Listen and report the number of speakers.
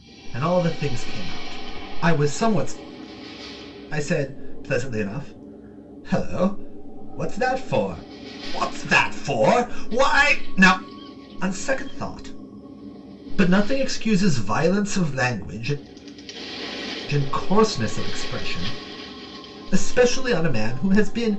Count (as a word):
one